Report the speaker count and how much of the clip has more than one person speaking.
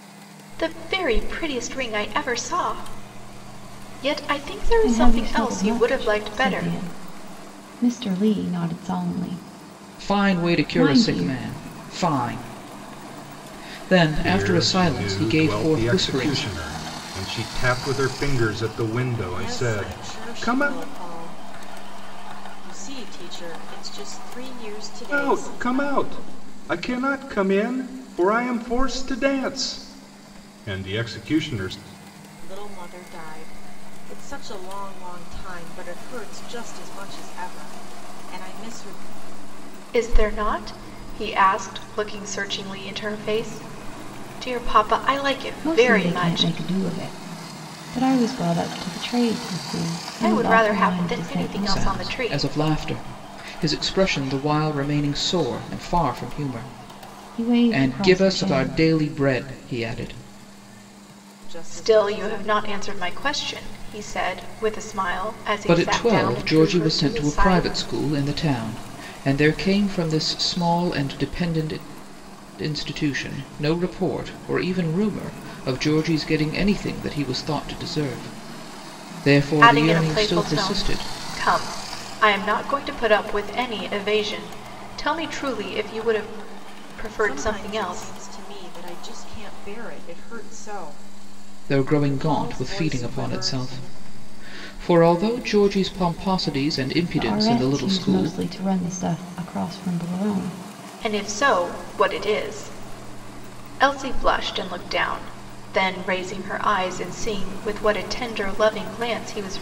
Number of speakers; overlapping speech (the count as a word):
five, about 20%